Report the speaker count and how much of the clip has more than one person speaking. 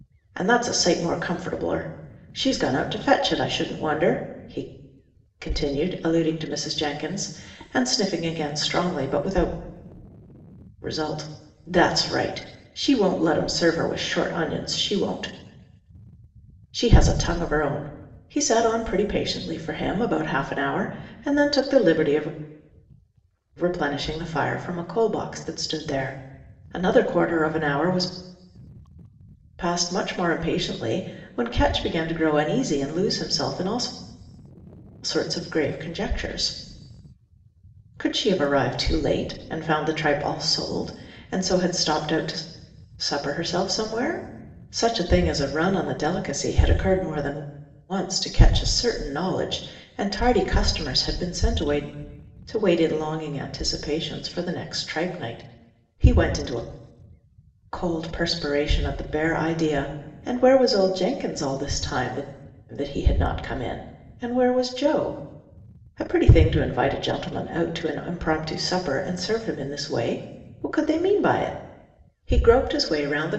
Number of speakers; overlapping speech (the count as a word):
one, no overlap